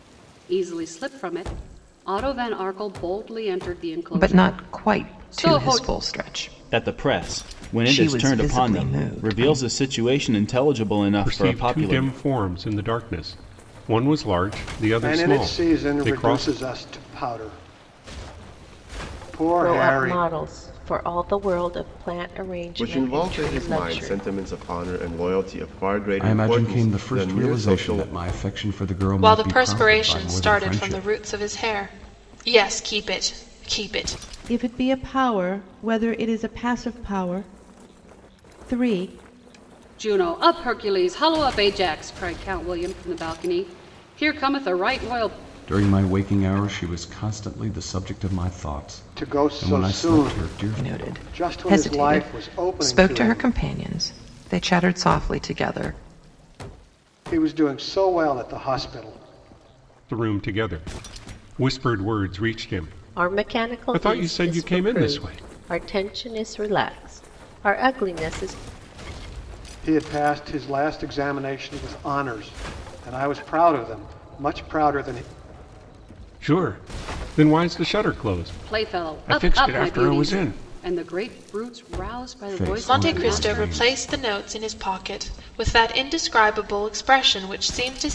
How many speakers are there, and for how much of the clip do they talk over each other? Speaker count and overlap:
10, about 27%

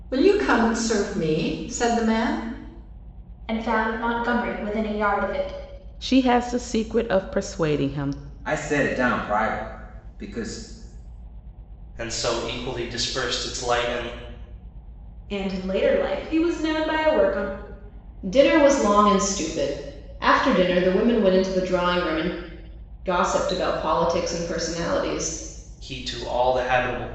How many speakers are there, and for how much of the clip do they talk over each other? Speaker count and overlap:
7, no overlap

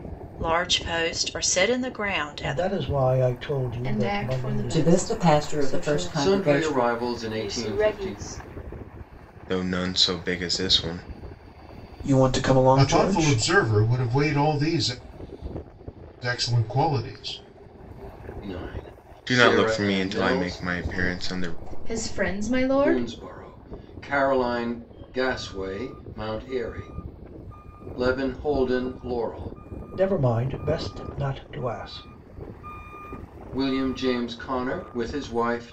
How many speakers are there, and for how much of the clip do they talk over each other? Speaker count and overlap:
9, about 21%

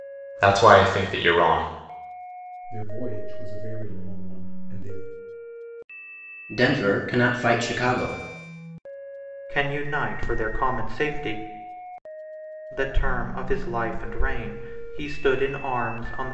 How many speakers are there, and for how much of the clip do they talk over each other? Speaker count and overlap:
4, no overlap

